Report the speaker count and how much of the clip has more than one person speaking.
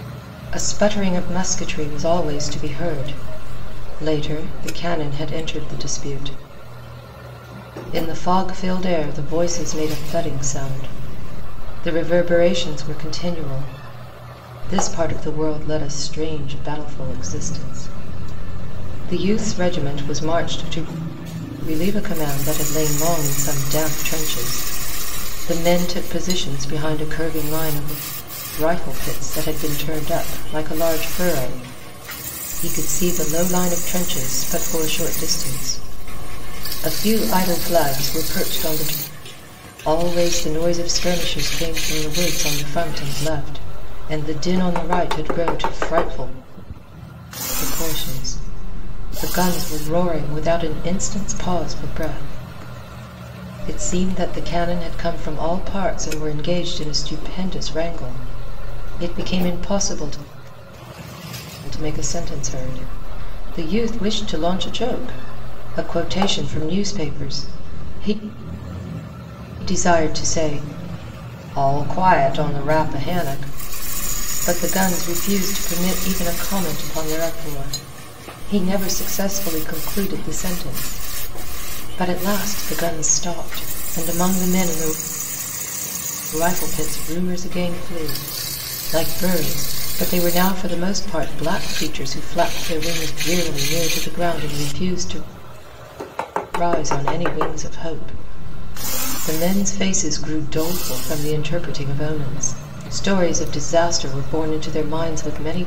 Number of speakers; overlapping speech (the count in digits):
1, no overlap